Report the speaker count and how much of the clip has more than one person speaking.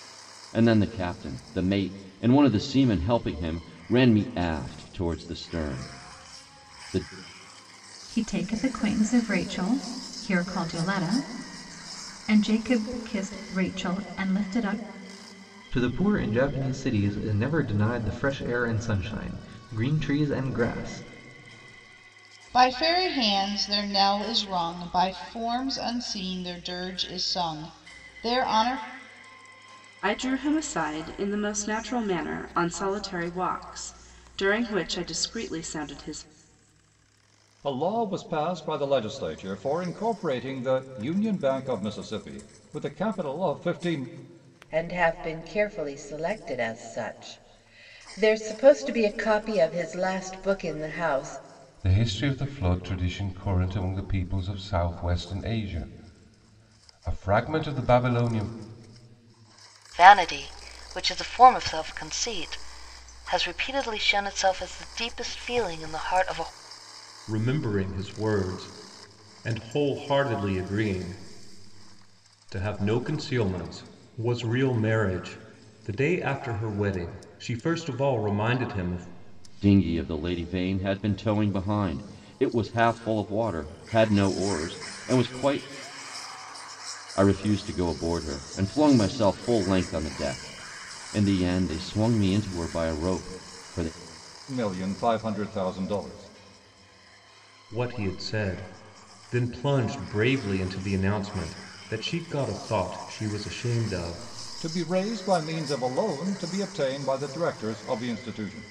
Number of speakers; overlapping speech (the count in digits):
10, no overlap